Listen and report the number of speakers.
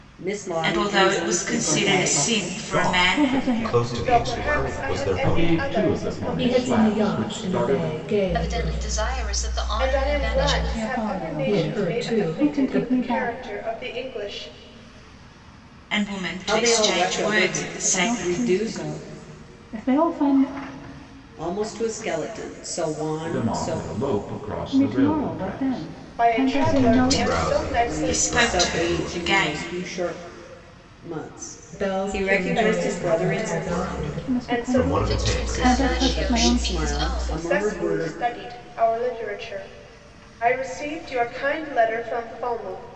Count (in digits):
9